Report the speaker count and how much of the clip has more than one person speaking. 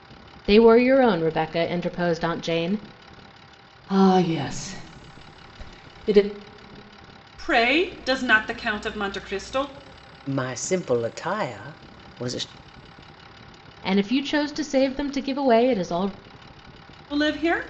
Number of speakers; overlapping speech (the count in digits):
4, no overlap